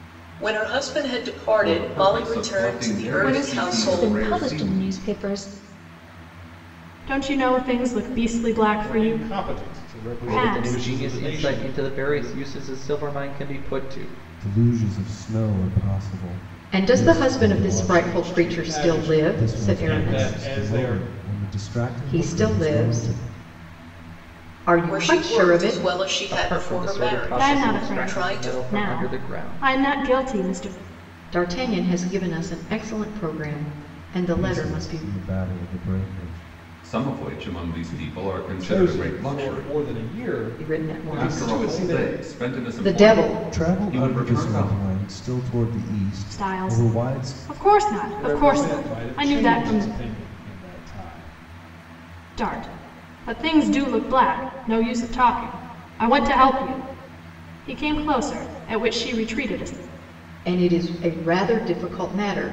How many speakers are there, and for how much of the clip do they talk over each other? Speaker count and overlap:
8, about 44%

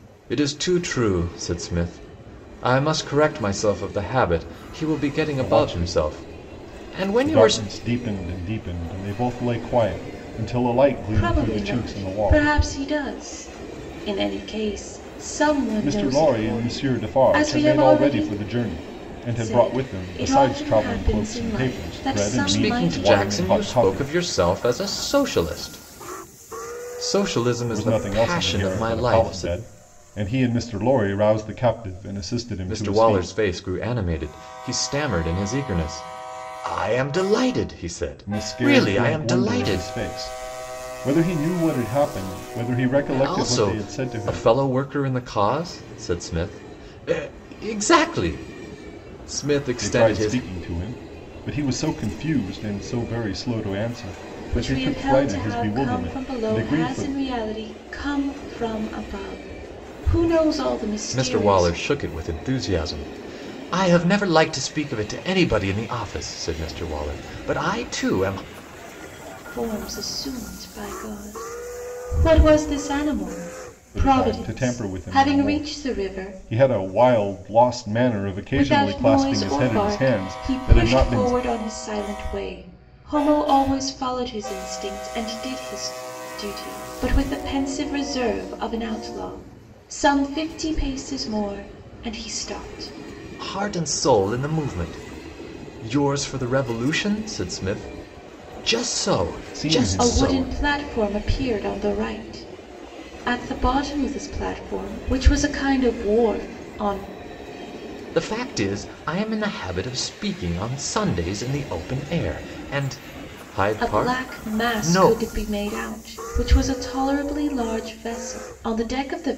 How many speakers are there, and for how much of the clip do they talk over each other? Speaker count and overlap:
3, about 24%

